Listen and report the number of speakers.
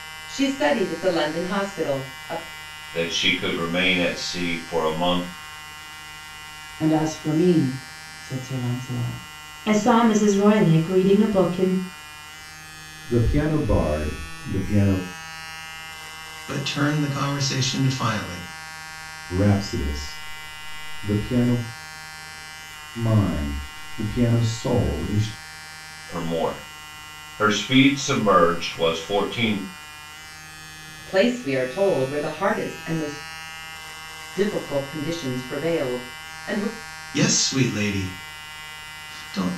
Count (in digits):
6